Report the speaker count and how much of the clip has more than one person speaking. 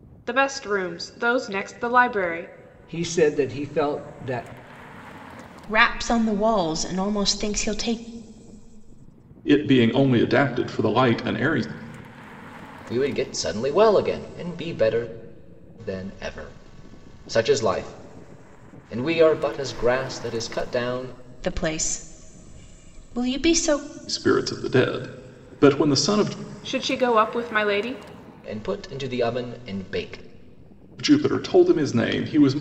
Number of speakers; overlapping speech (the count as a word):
five, no overlap